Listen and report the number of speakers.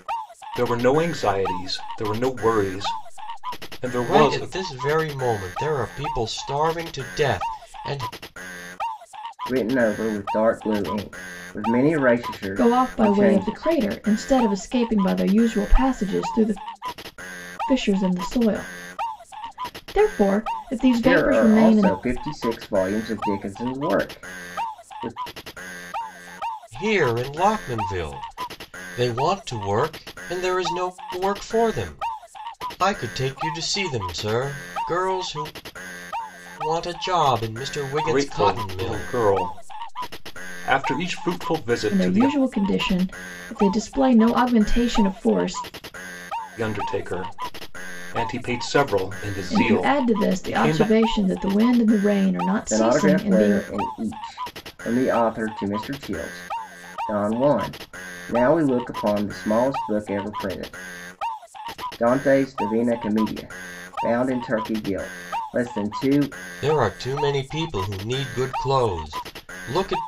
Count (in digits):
4